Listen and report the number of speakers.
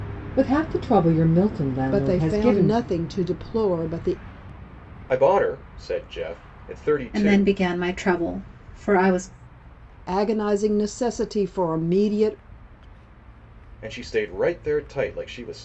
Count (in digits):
4